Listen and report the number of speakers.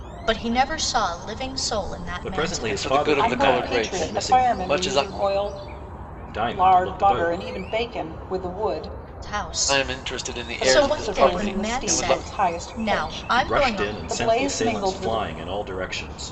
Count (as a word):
four